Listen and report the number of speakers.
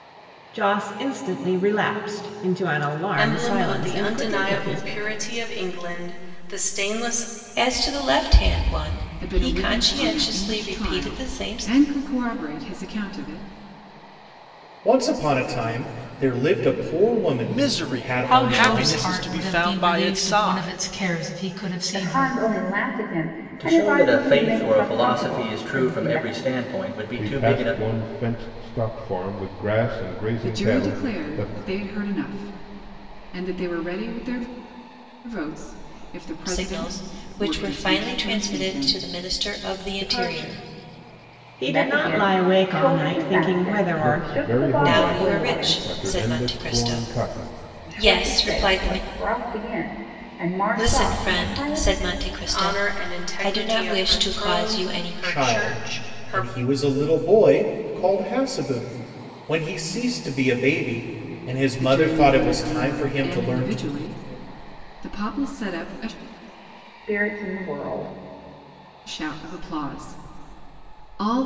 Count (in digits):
10